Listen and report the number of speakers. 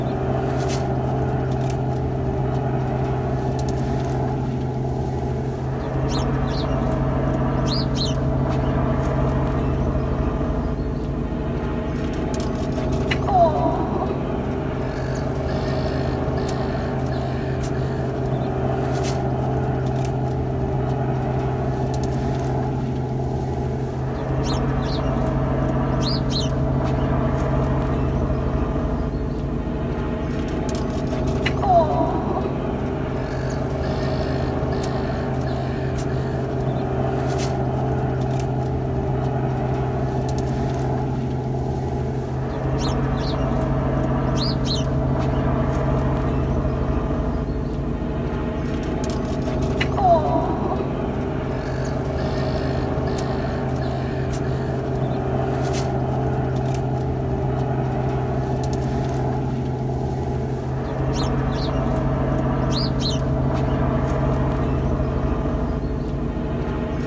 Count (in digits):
0